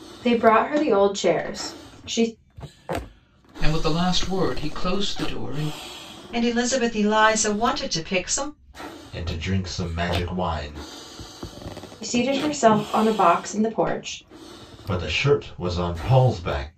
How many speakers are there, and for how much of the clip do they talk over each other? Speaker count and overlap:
four, no overlap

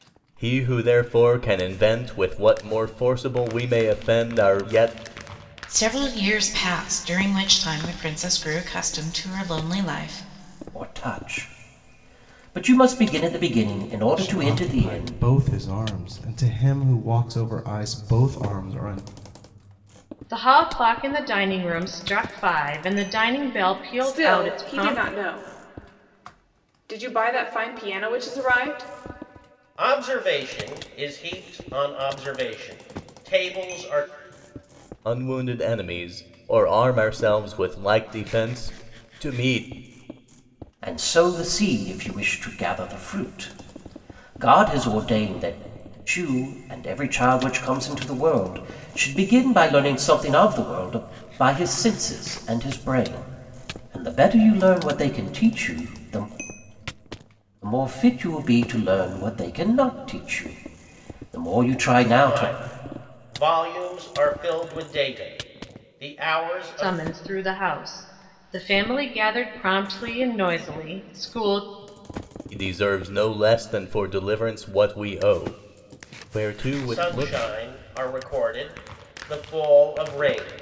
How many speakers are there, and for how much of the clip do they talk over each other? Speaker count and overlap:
seven, about 5%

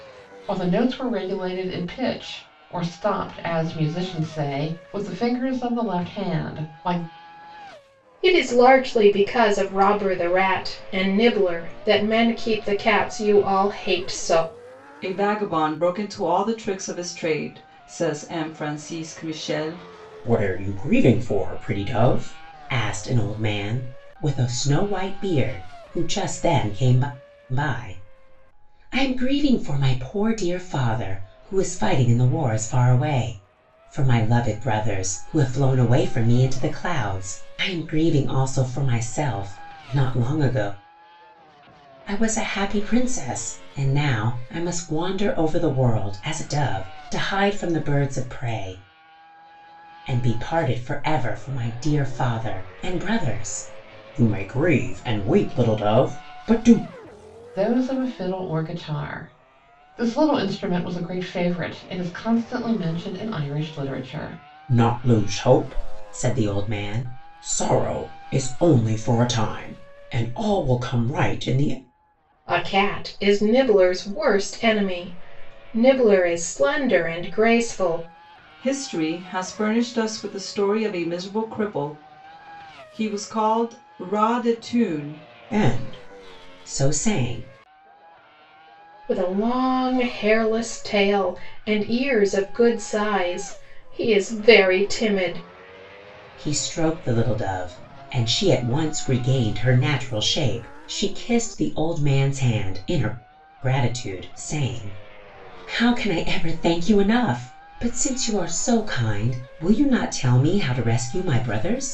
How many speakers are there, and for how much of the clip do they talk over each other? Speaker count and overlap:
four, no overlap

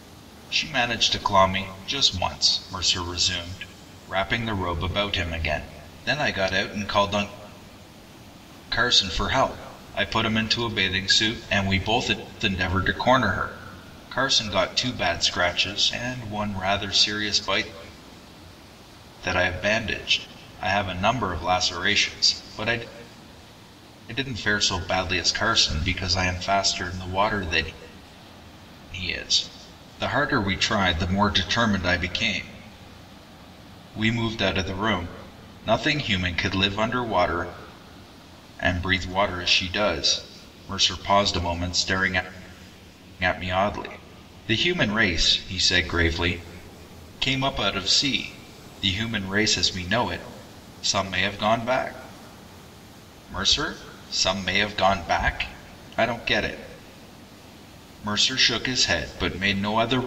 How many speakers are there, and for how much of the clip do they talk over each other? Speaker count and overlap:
one, no overlap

